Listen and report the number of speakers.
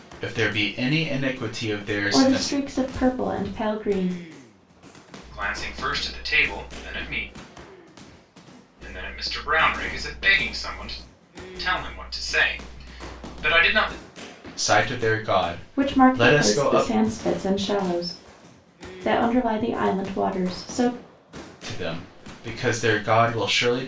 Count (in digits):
3